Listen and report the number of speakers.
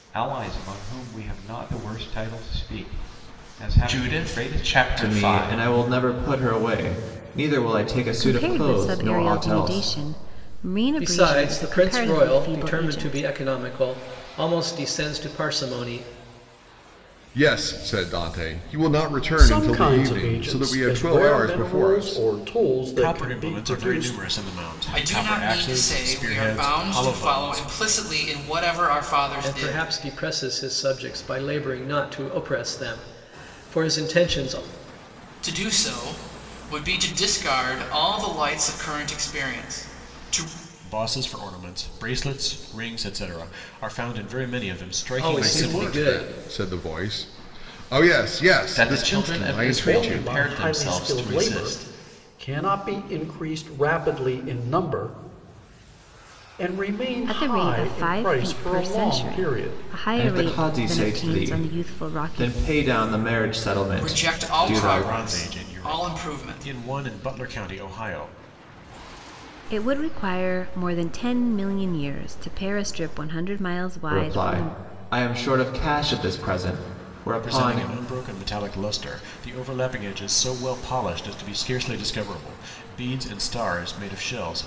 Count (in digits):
9